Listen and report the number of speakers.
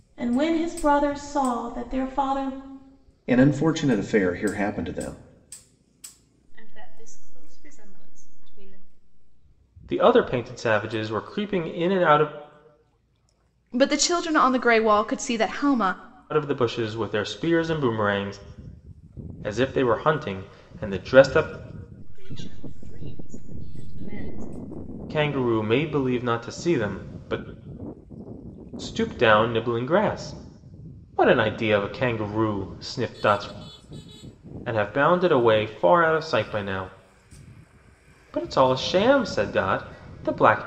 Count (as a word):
five